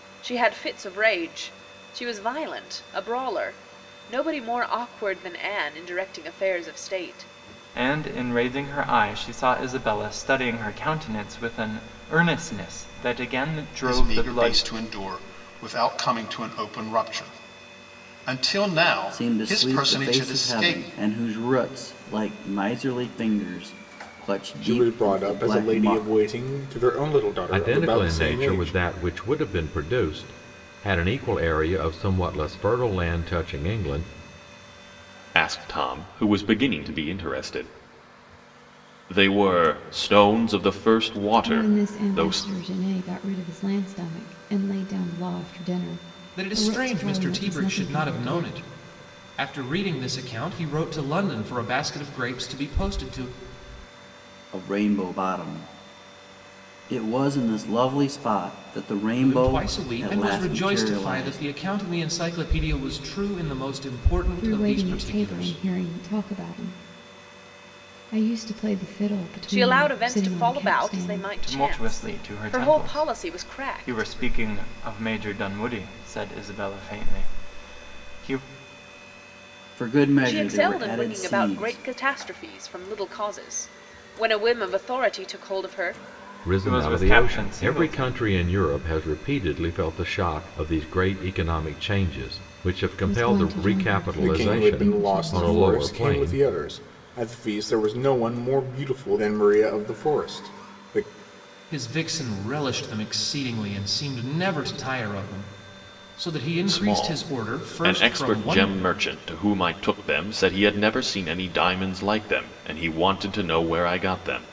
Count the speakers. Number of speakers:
nine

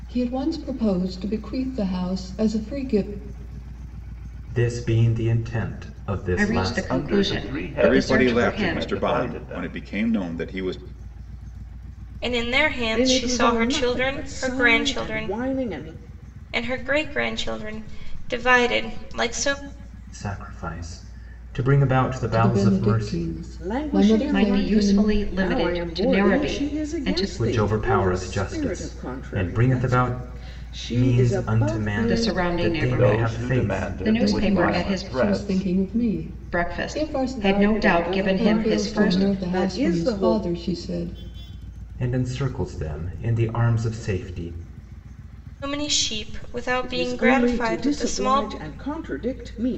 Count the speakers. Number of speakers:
seven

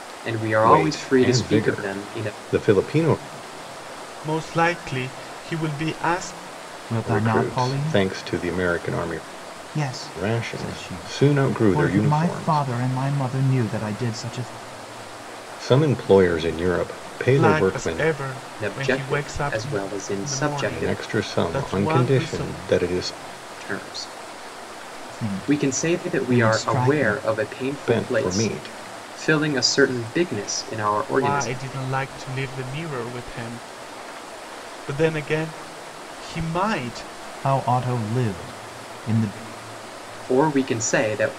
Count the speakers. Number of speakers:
four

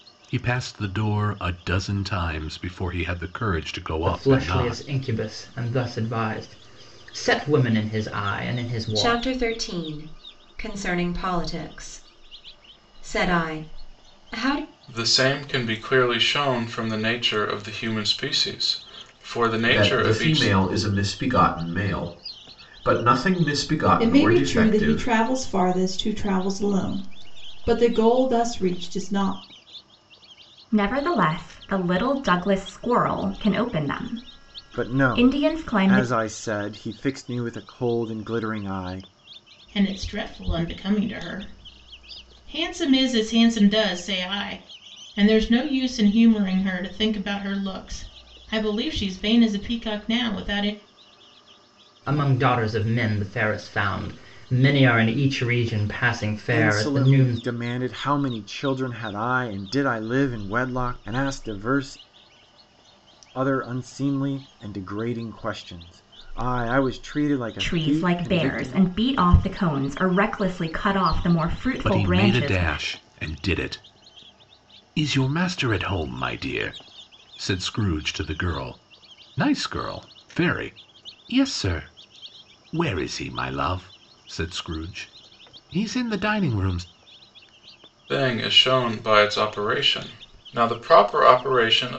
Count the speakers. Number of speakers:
nine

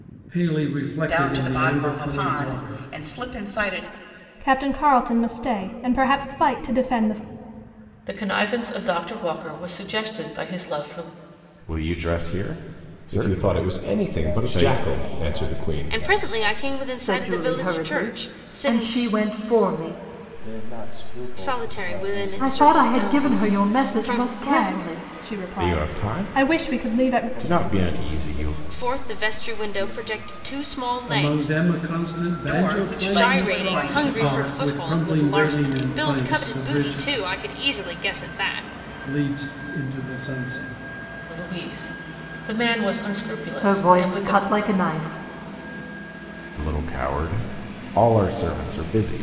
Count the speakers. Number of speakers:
nine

